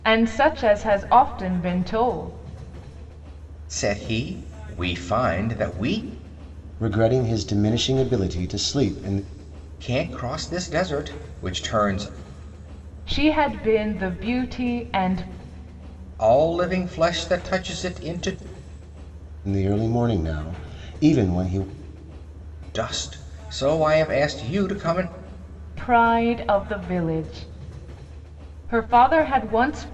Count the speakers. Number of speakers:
three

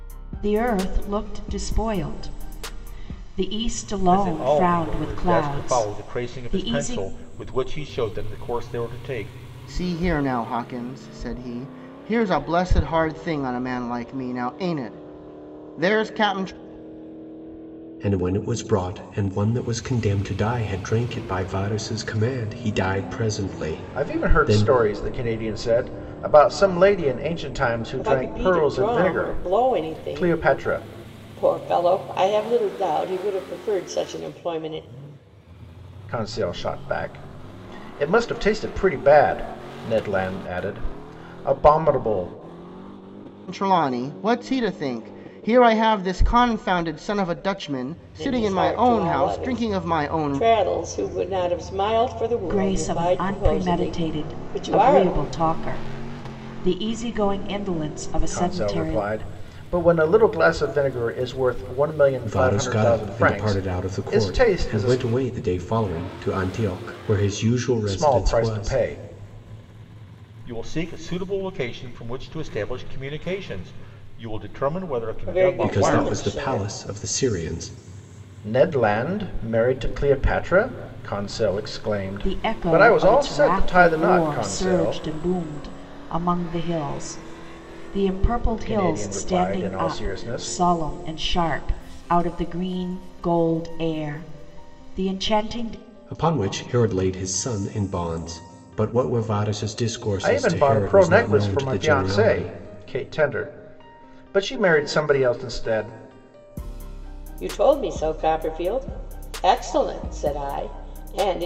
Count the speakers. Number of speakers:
six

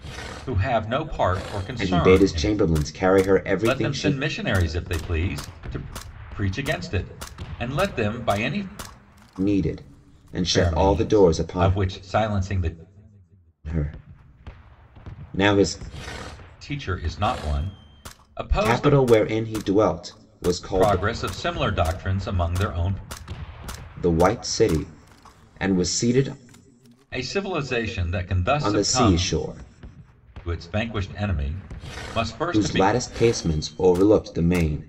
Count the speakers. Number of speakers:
two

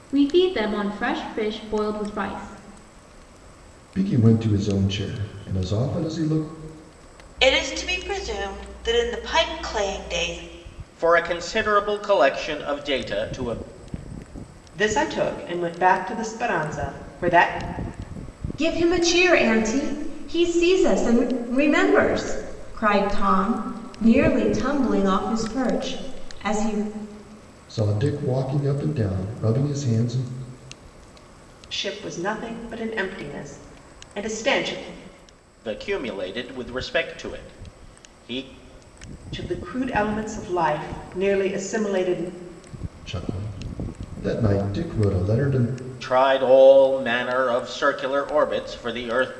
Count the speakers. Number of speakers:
six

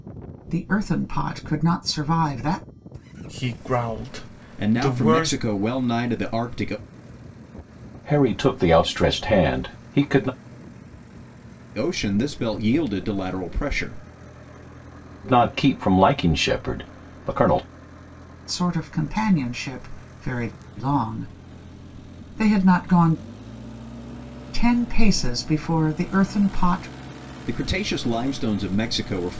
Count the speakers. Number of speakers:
four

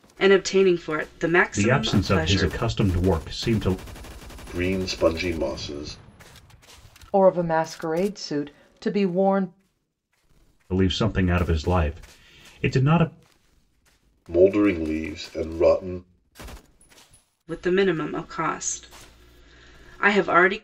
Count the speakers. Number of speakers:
four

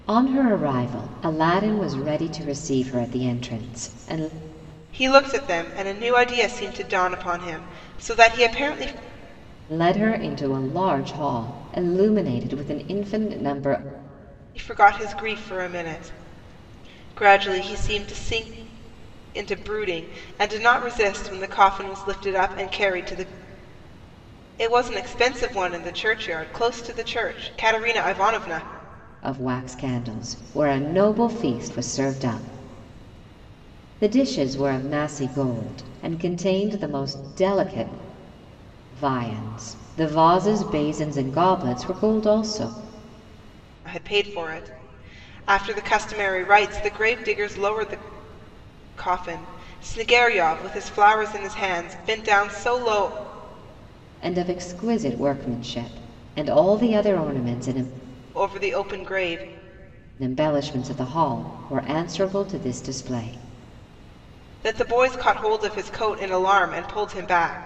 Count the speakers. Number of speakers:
two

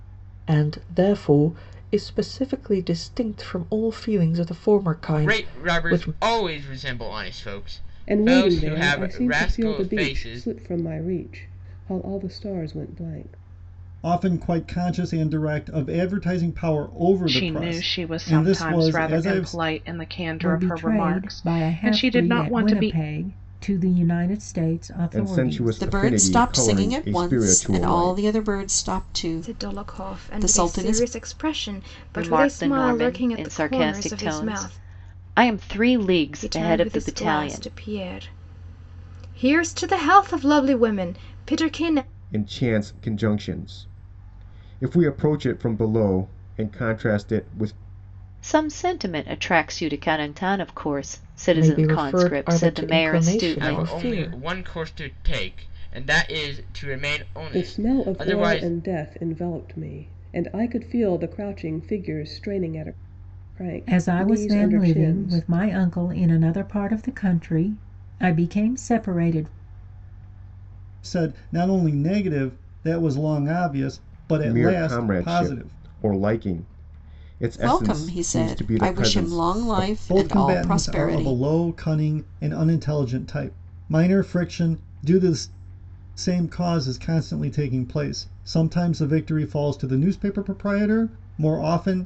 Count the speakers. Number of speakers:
ten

